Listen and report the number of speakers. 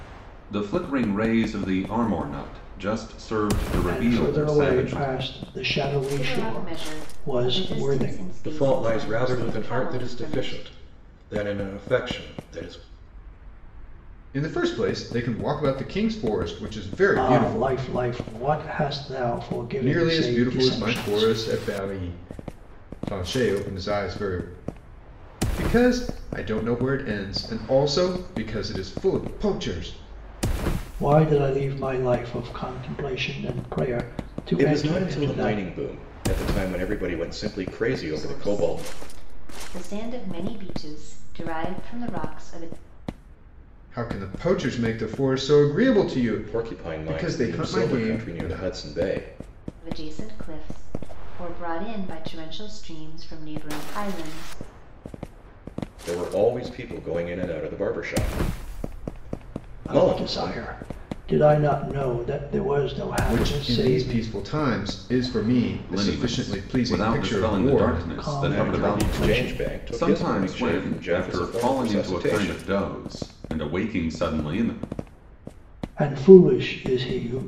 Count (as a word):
five